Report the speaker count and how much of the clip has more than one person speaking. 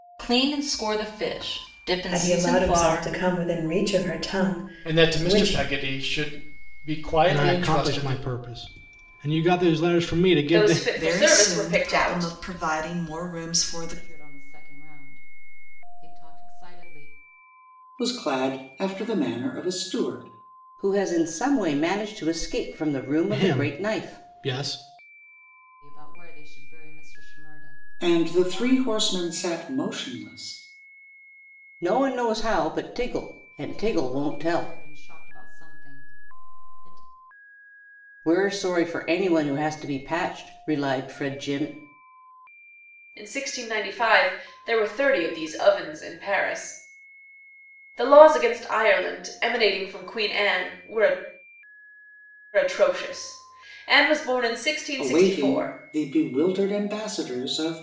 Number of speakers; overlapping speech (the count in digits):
9, about 16%